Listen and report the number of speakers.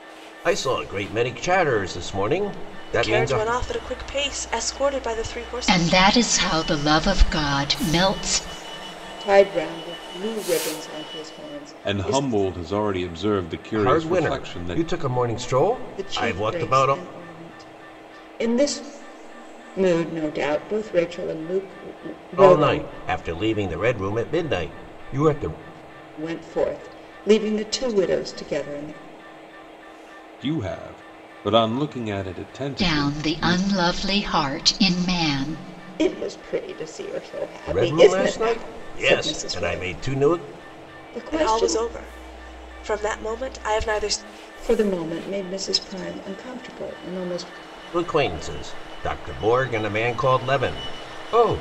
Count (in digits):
5